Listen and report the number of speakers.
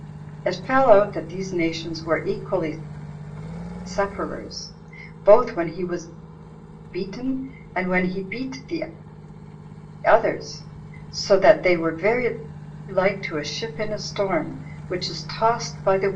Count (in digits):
1